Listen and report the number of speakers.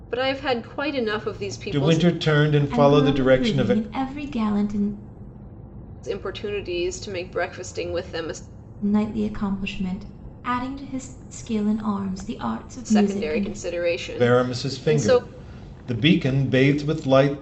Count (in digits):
3